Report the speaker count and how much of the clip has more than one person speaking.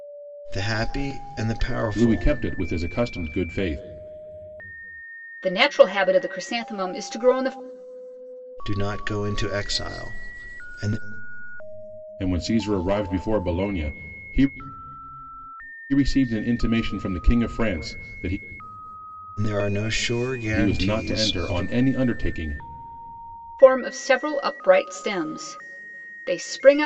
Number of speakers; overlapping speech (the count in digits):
3, about 6%